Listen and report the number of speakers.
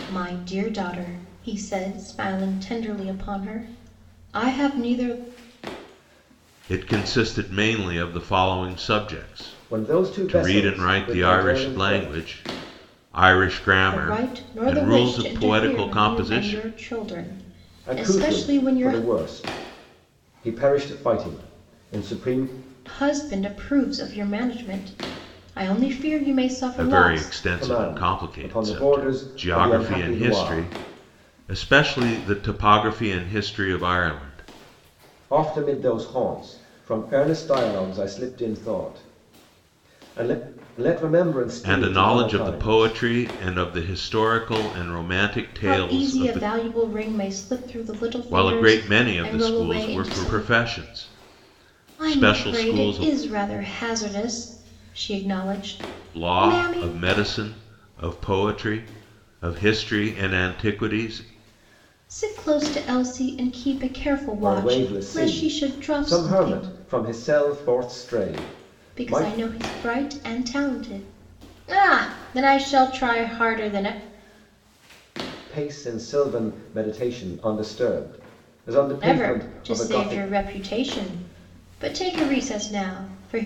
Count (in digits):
3